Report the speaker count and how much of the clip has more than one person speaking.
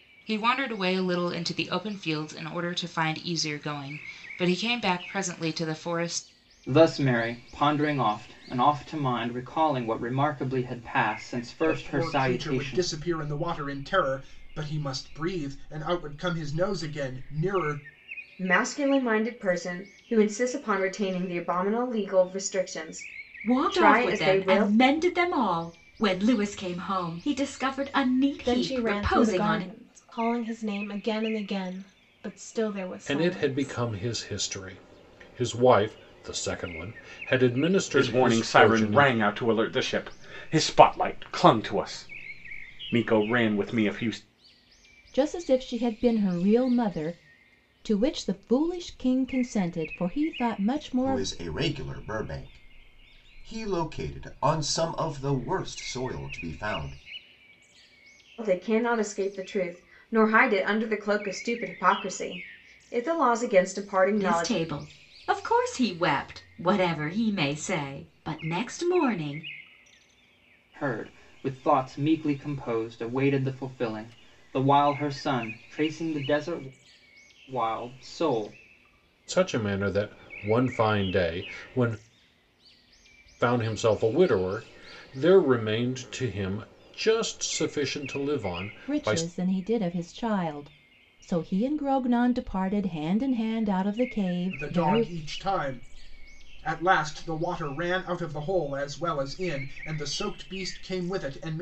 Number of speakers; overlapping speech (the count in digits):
10, about 8%